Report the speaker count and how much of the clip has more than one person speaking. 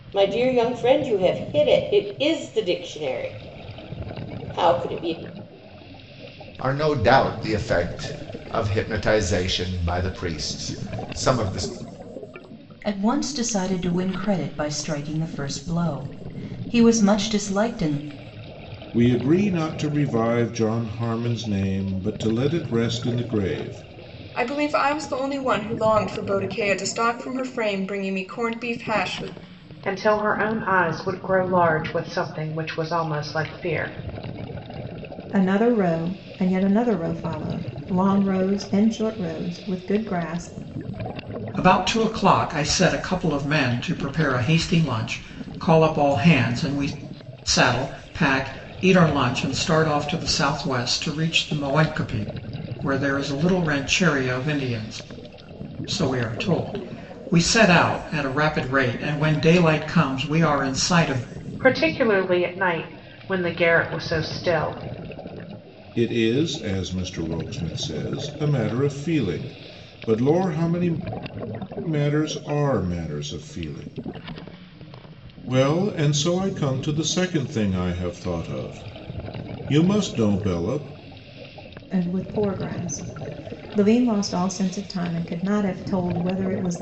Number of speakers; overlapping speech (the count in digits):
8, no overlap